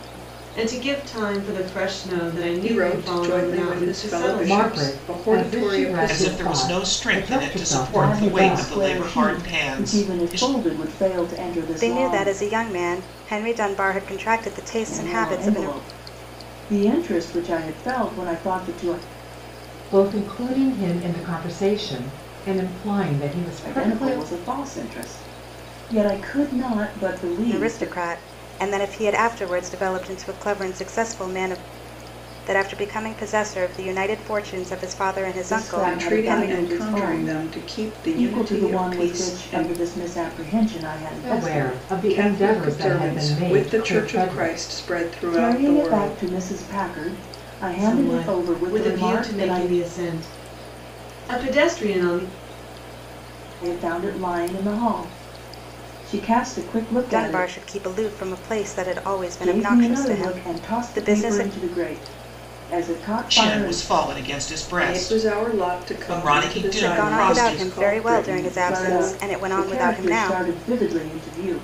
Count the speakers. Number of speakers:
six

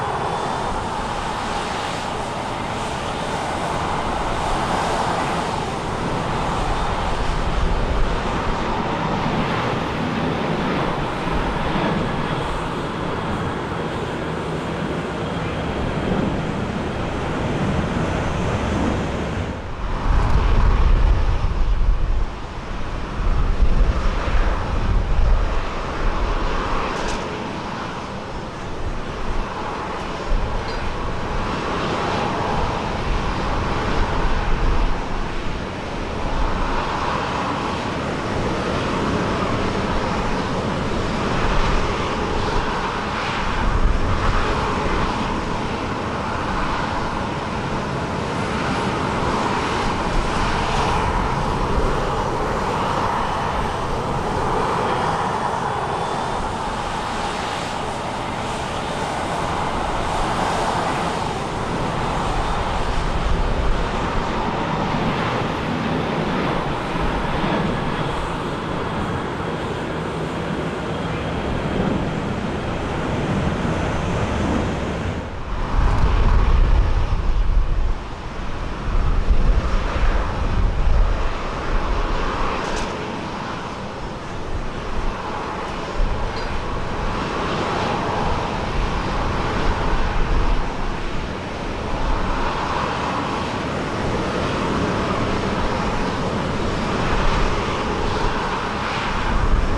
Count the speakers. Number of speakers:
zero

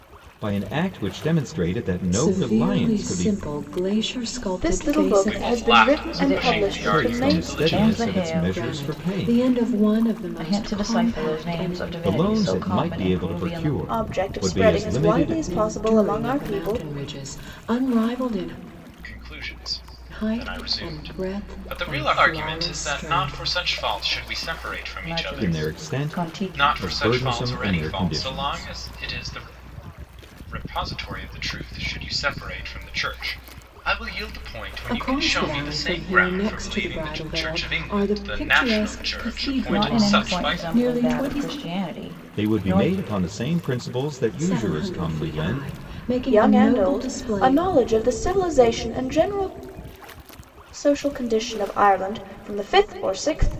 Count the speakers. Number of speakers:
five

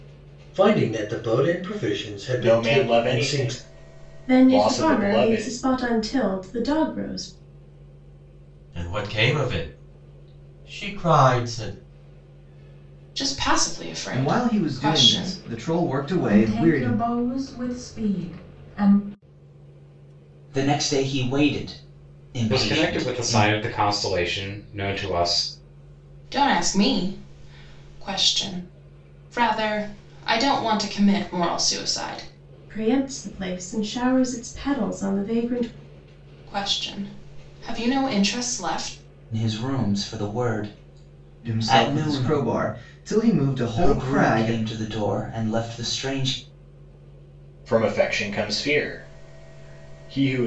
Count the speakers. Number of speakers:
nine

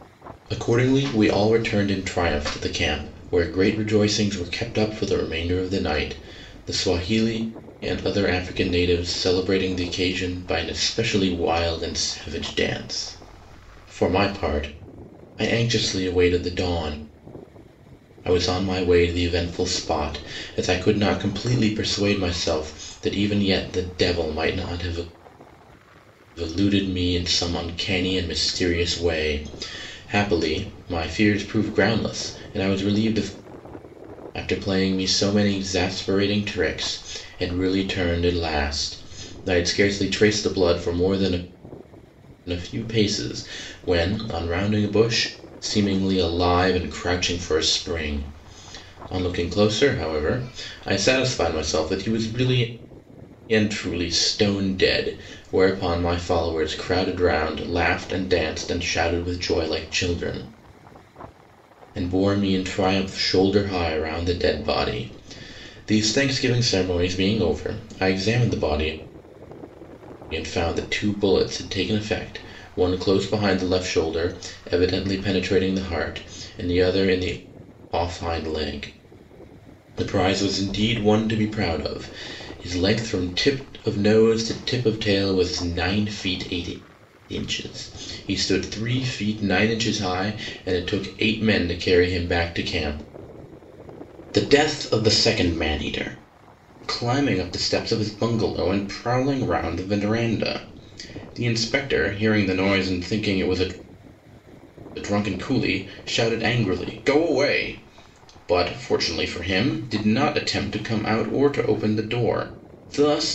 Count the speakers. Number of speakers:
one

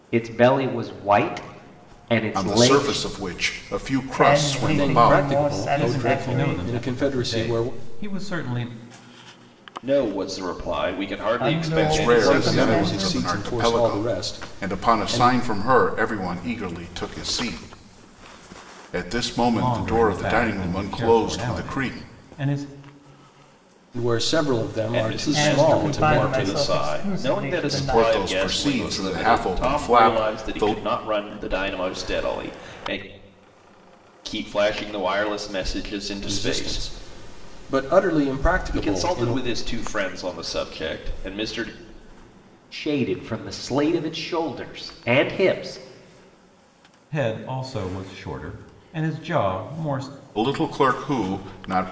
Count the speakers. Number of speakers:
six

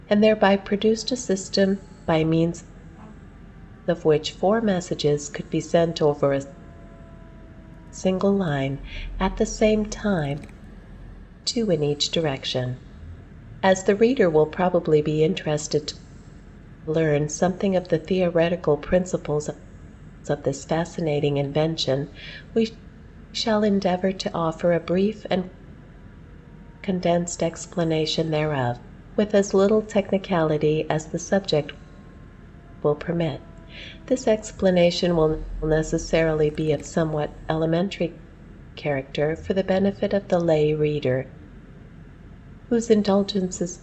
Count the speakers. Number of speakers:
one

